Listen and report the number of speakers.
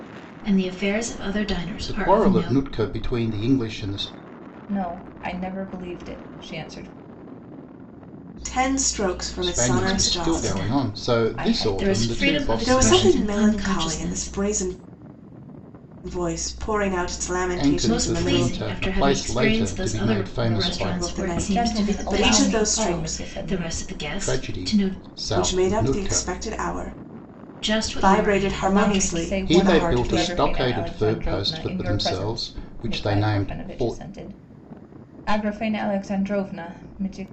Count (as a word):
four